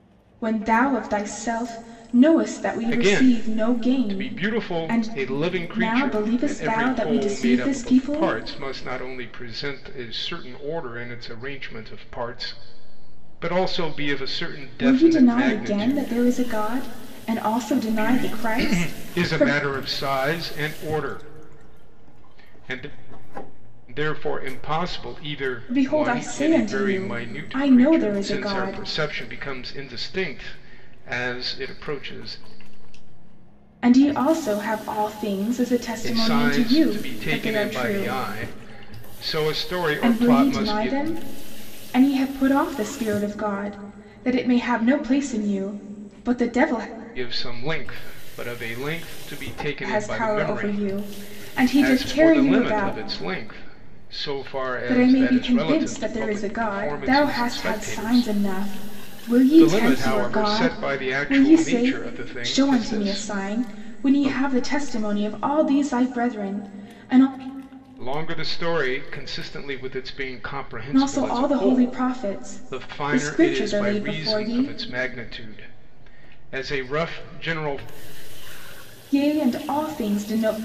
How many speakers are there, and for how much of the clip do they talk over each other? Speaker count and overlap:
two, about 36%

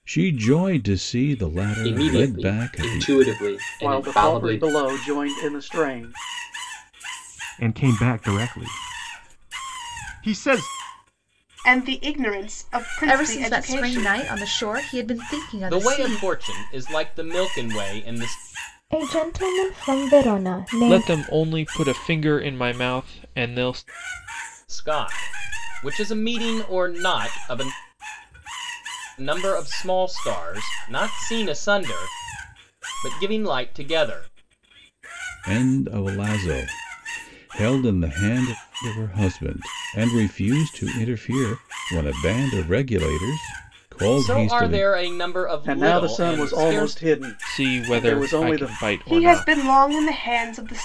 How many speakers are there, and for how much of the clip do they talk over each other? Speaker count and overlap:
nine, about 16%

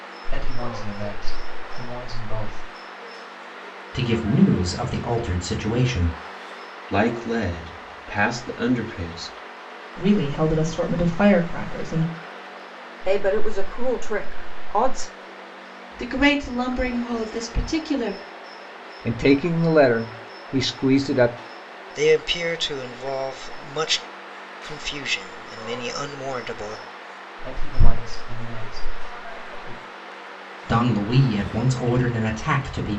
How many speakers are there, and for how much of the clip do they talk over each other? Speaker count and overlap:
eight, no overlap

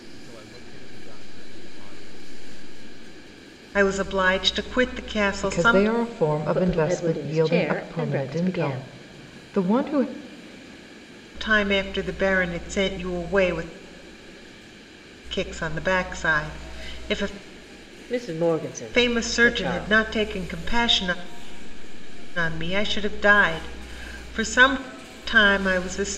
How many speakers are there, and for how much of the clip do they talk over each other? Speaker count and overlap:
four, about 20%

